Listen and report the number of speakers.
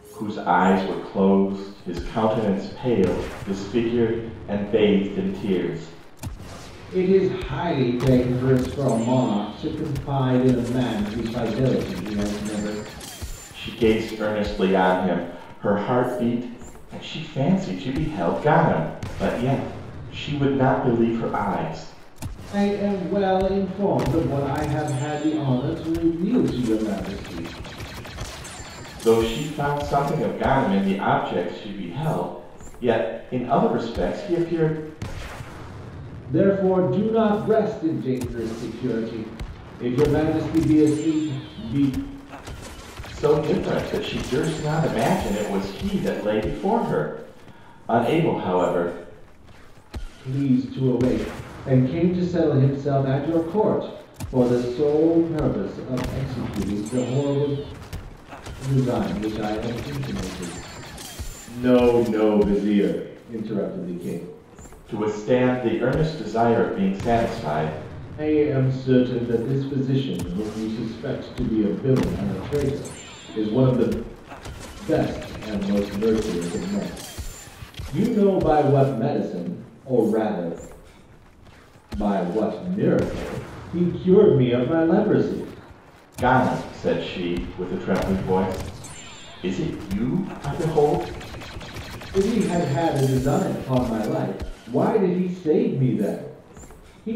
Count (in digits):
2